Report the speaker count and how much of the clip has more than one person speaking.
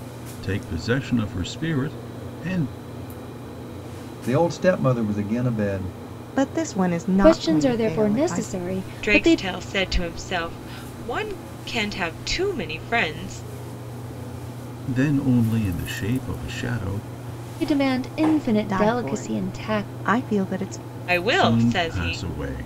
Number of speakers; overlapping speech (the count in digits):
5, about 18%